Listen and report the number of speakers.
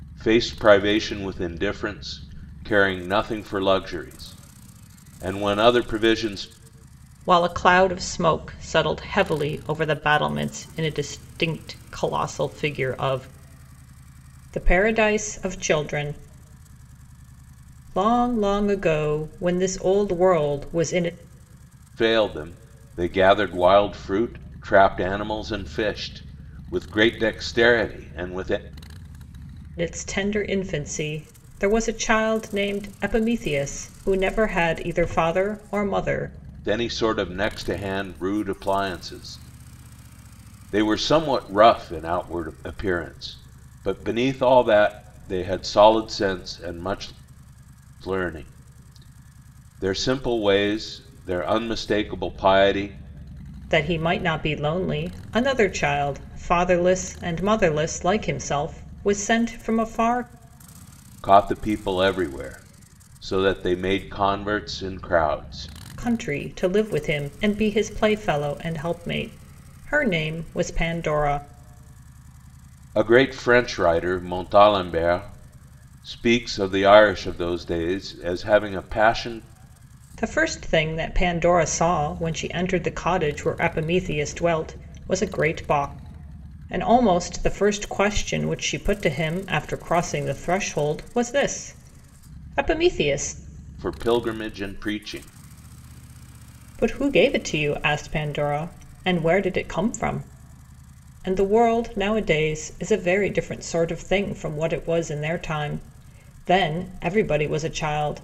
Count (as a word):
two